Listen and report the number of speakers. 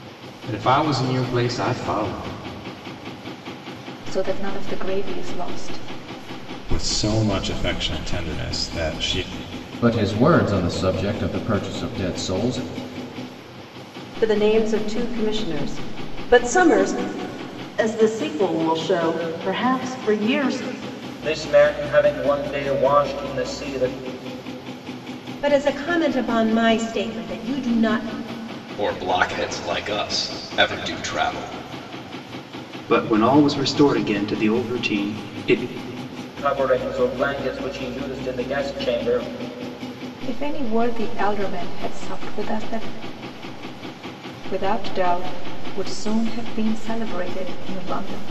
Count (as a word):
ten